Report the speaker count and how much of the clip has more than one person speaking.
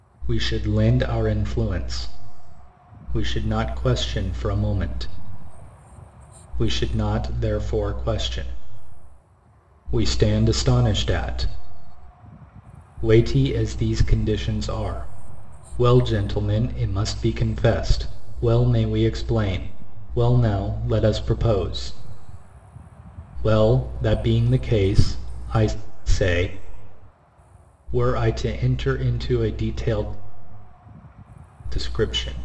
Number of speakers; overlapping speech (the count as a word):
one, no overlap